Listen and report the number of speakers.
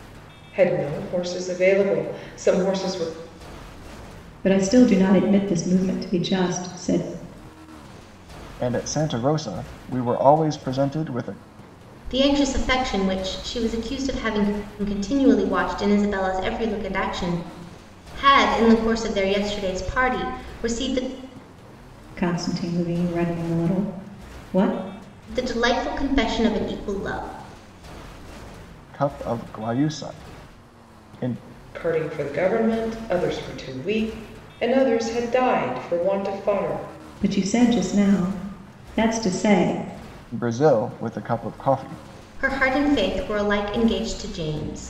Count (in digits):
4